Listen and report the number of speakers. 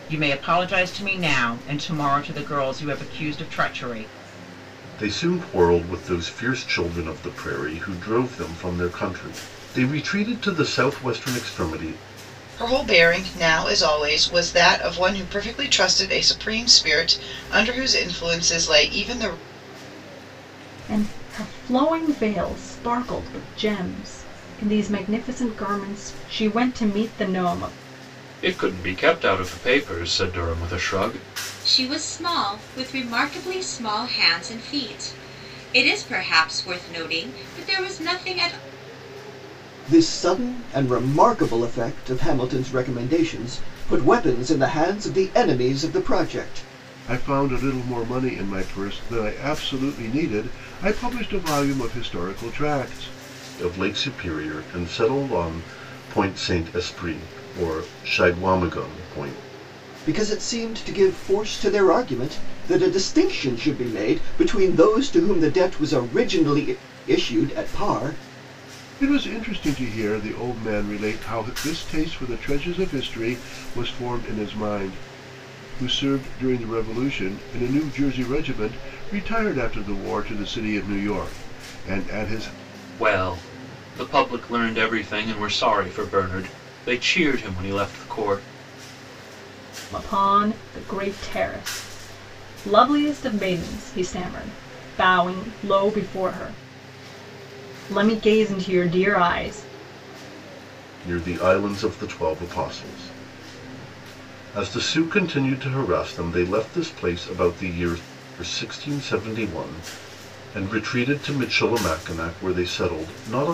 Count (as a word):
eight